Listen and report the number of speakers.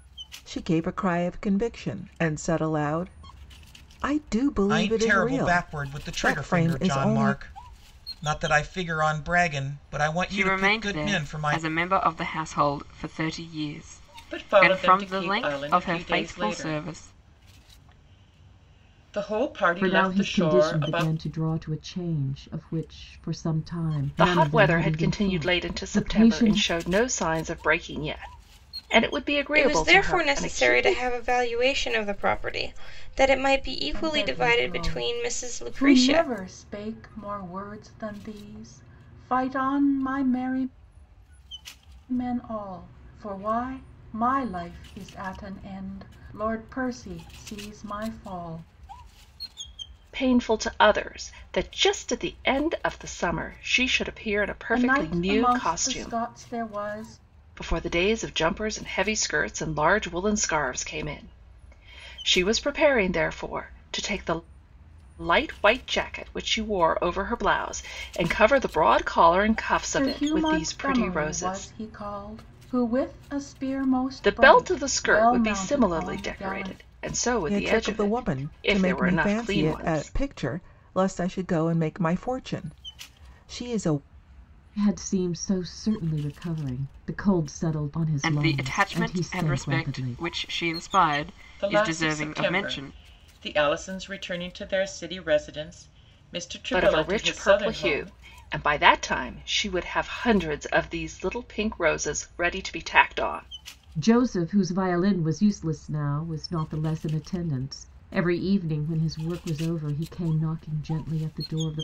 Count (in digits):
8